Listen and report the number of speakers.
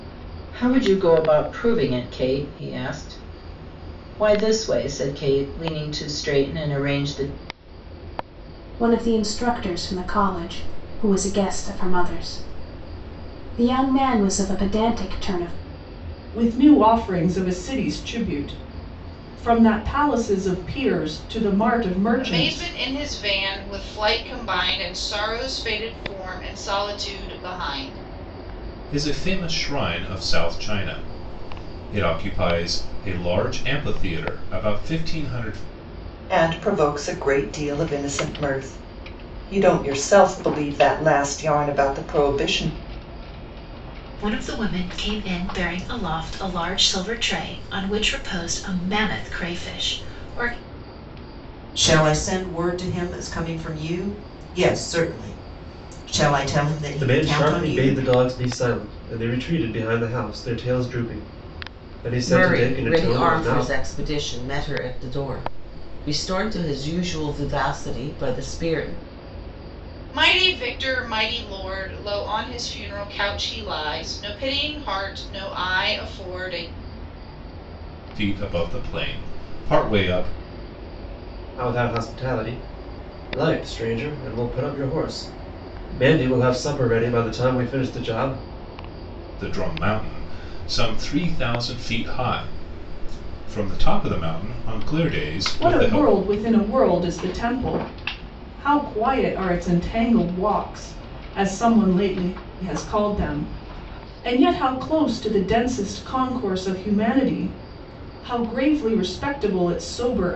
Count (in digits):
10